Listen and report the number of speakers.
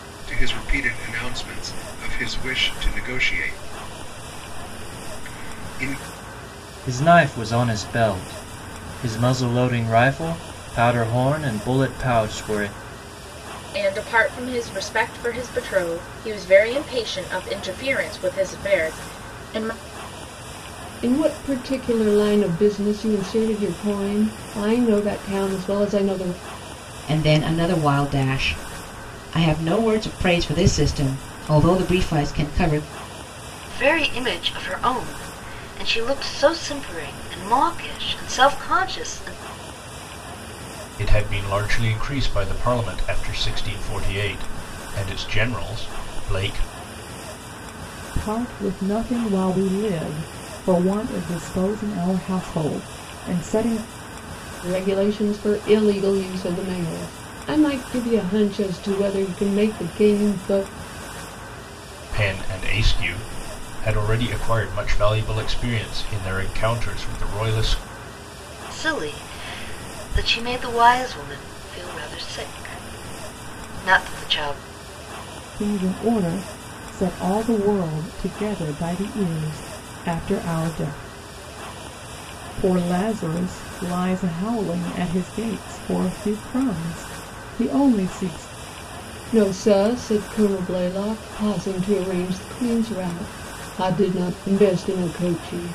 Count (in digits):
8